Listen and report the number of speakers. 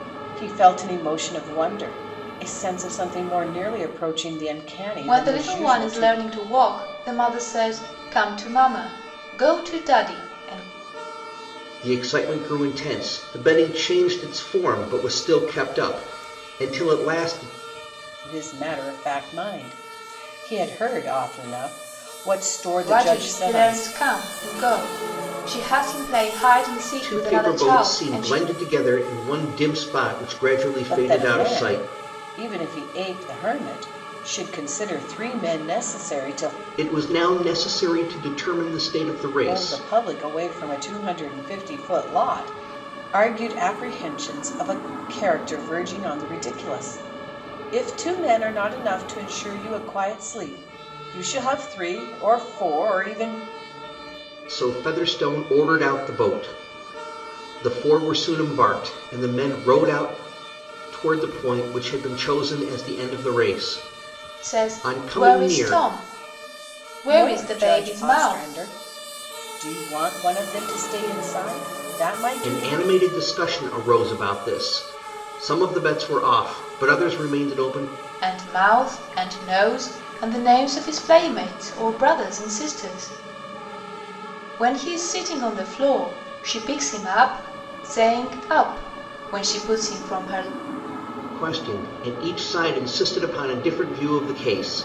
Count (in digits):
3